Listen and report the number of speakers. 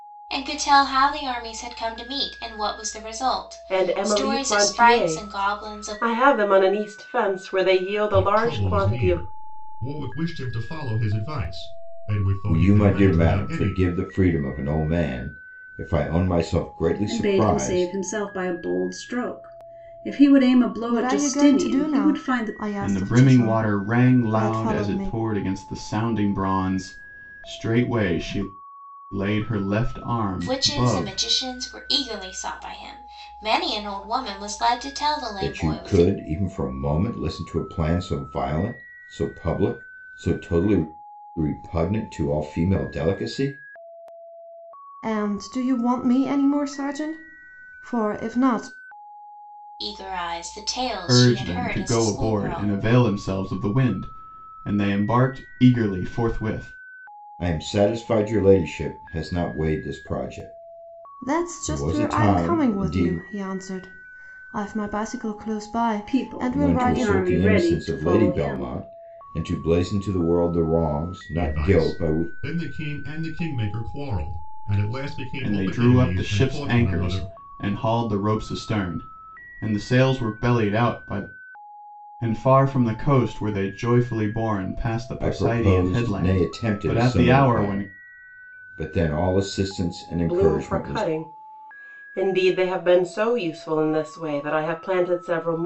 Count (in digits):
7